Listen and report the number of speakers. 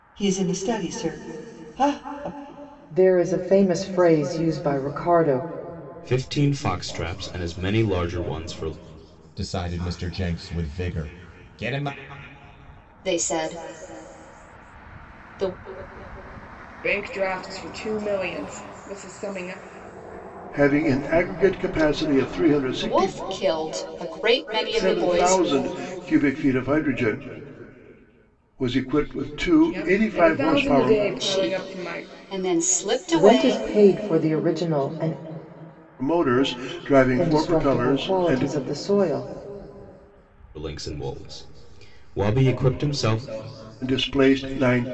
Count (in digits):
7